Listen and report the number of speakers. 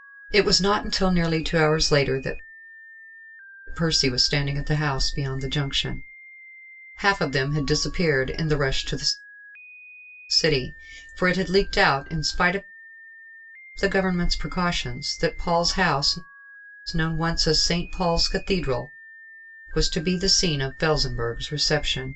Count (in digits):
1